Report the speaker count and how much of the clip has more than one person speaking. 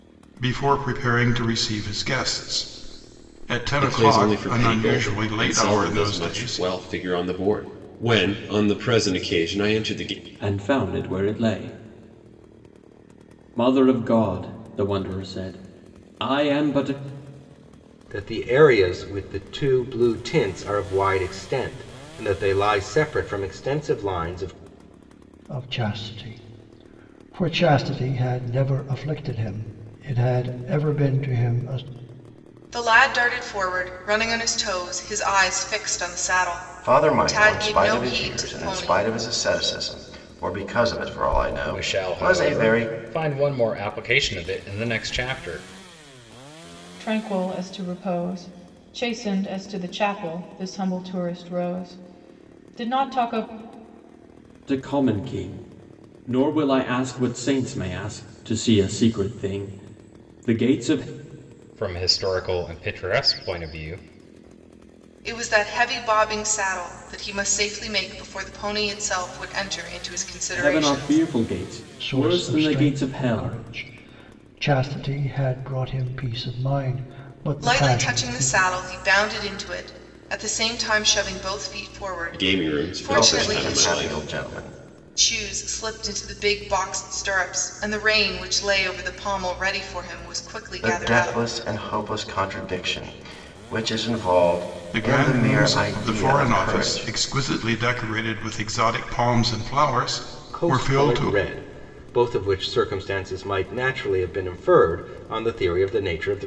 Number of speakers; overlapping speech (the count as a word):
nine, about 14%